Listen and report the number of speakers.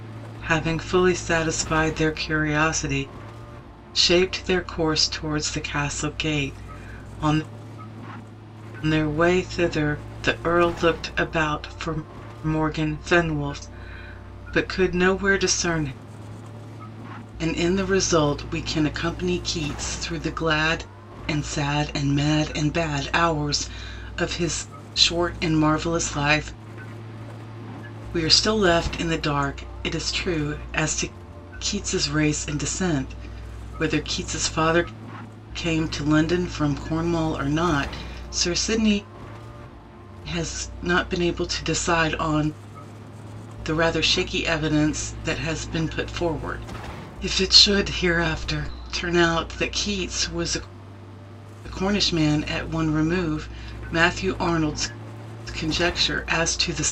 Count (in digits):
1